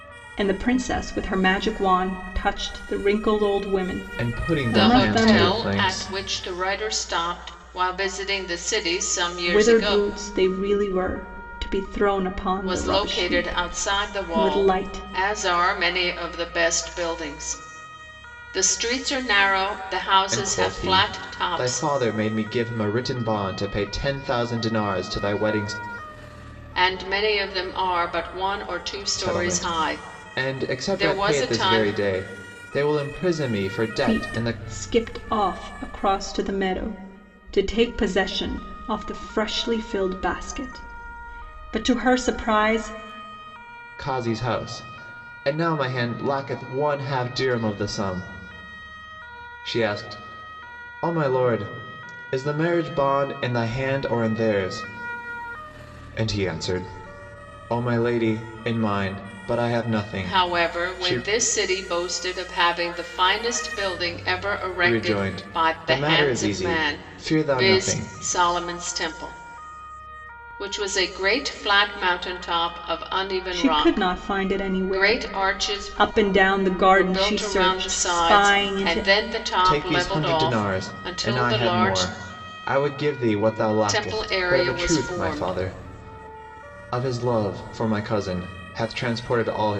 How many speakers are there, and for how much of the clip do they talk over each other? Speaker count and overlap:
3, about 26%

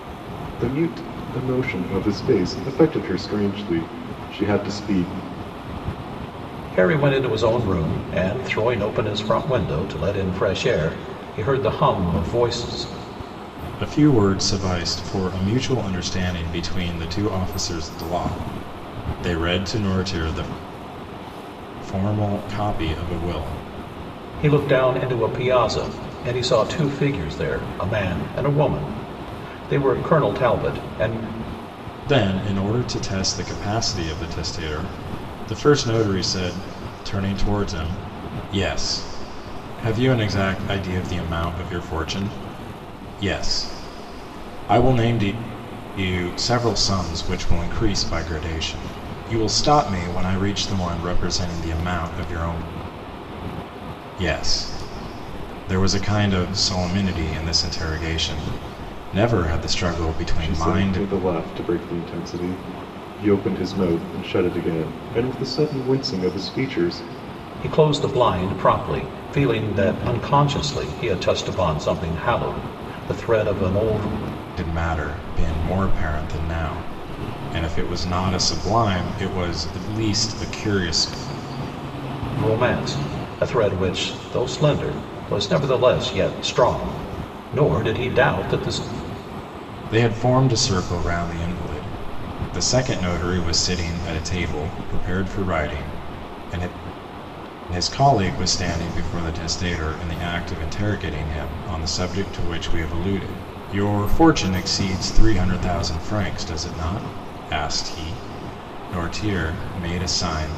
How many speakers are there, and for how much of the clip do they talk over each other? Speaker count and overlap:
3, about 1%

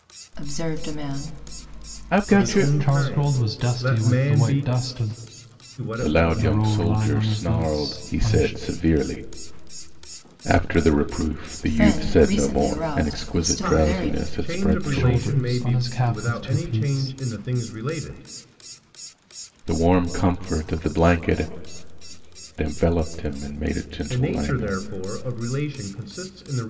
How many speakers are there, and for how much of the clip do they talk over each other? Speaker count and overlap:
4, about 42%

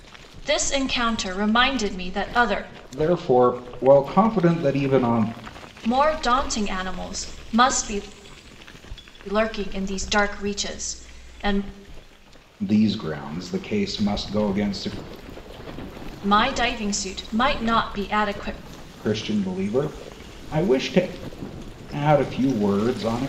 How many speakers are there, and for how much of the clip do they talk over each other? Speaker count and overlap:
2, no overlap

